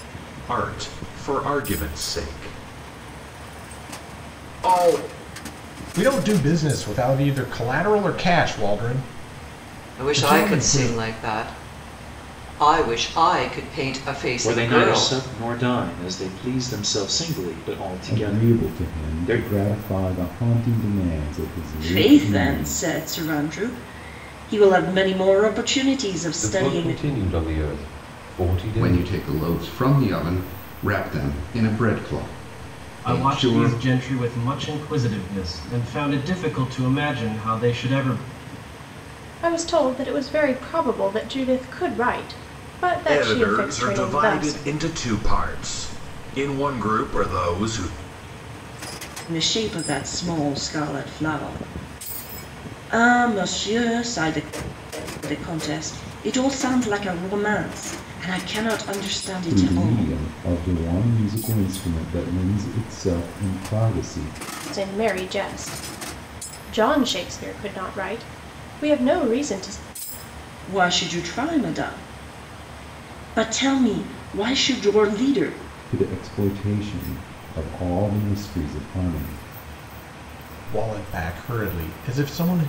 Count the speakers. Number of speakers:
ten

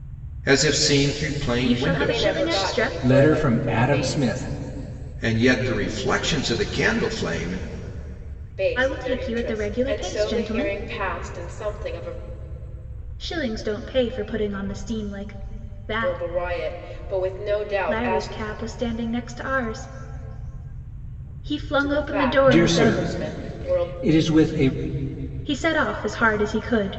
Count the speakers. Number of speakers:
four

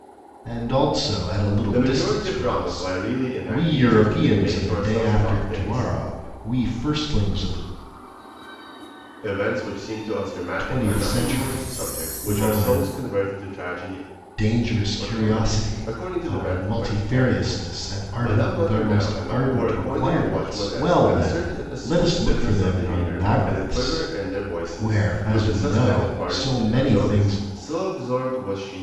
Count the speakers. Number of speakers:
two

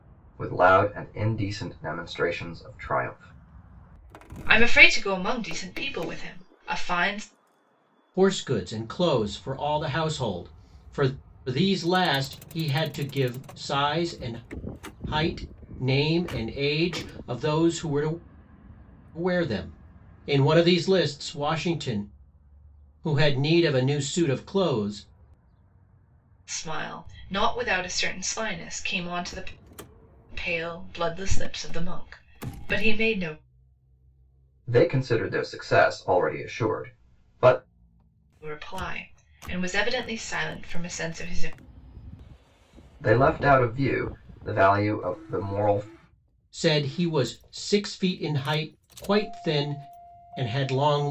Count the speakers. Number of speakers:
three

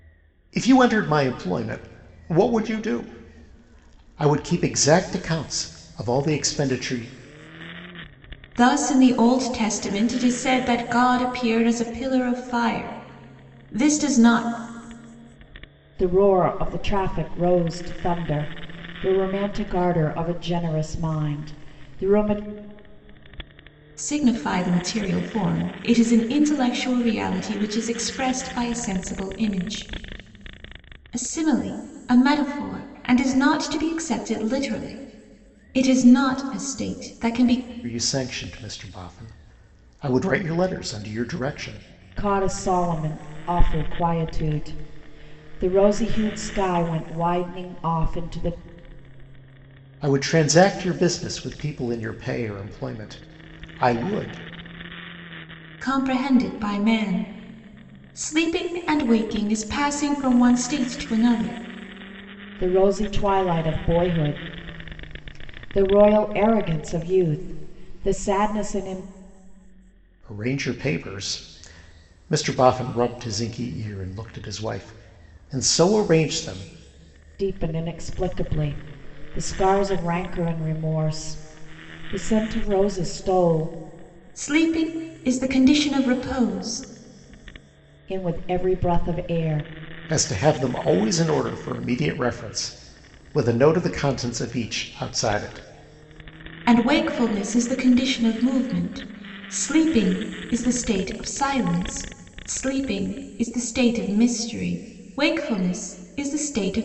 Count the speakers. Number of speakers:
three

